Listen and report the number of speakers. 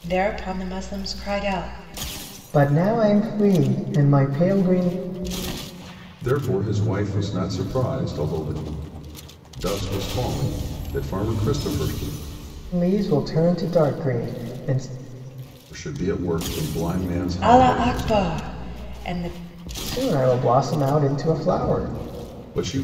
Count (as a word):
three